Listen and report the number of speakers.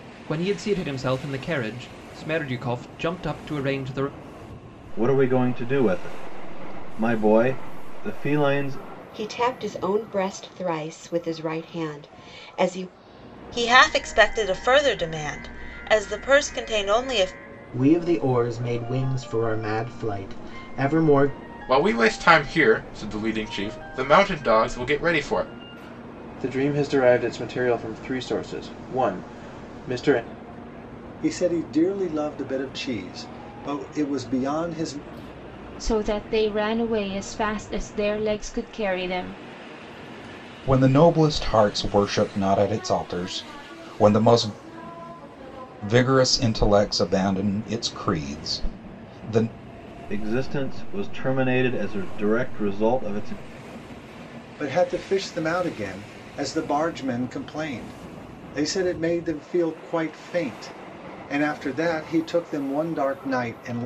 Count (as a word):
ten